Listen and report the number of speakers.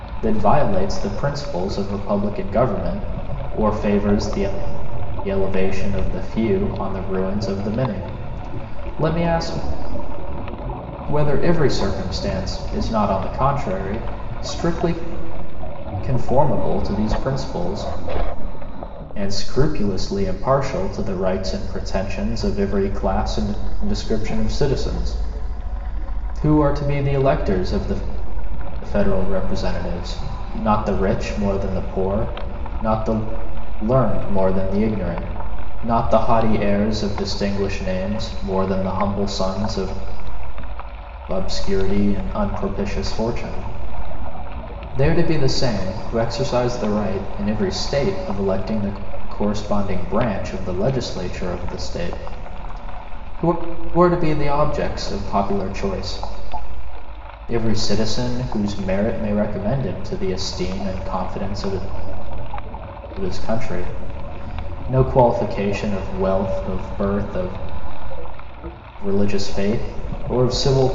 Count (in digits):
1